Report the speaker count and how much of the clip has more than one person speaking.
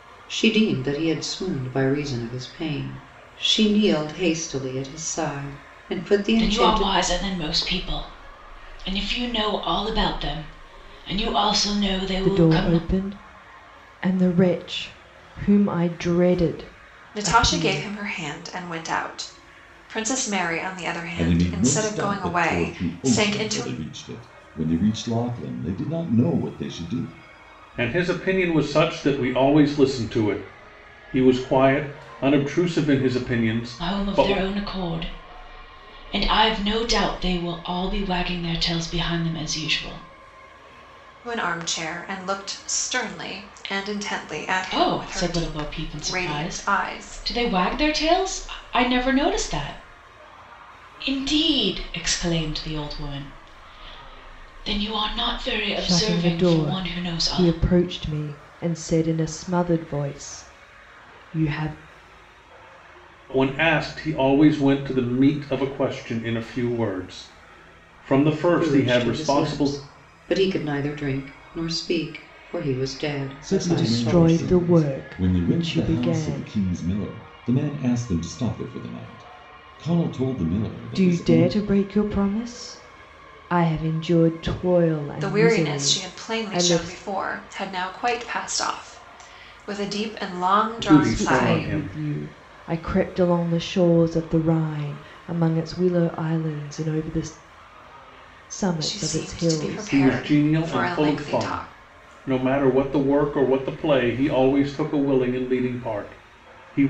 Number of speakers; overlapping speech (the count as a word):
six, about 19%